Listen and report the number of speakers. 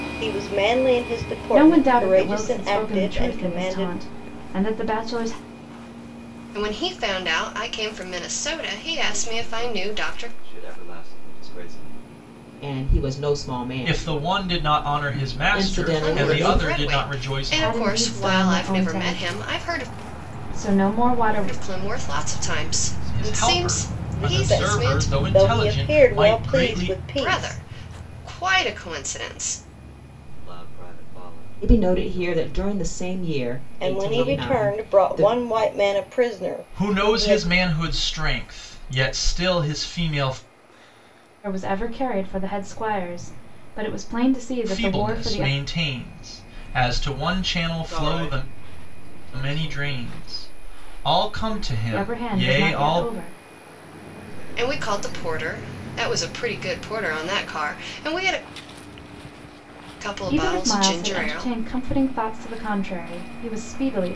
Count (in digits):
6